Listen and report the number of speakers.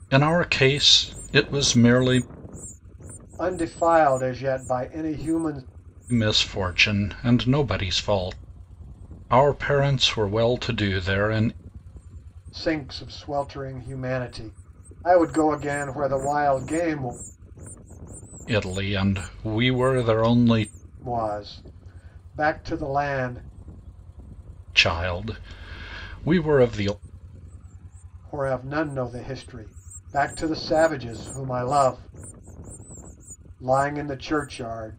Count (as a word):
two